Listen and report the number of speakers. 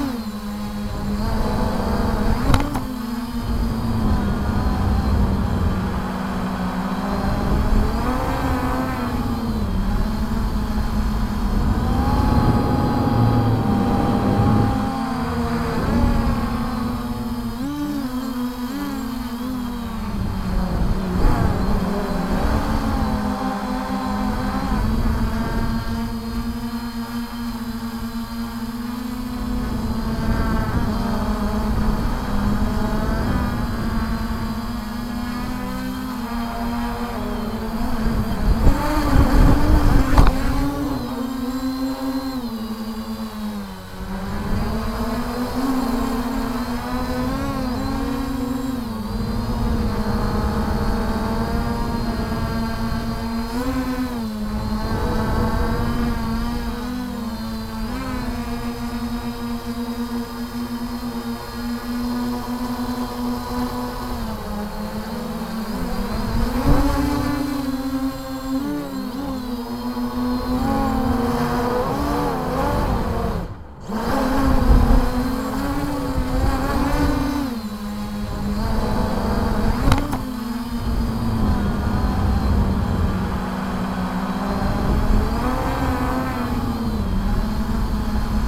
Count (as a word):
zero